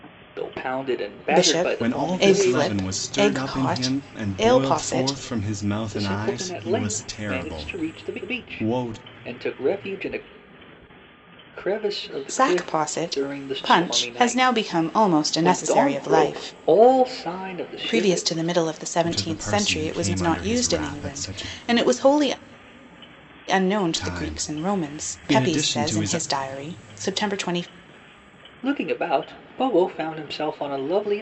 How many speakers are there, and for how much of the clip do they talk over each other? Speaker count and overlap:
3, about 53%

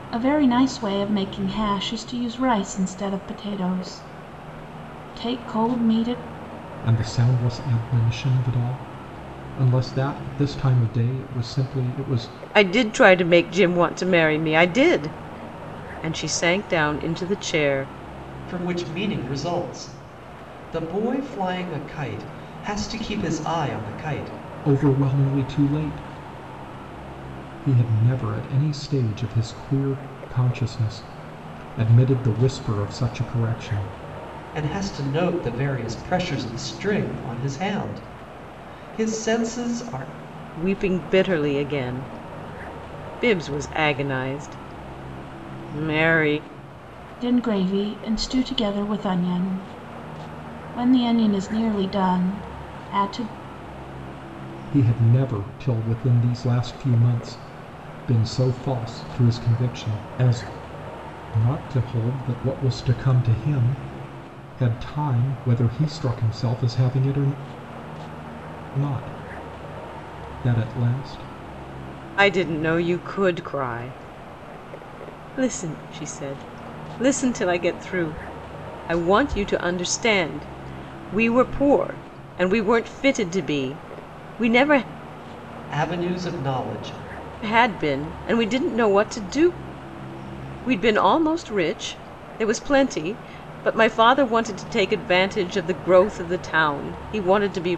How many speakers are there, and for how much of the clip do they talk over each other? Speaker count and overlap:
4, no overlap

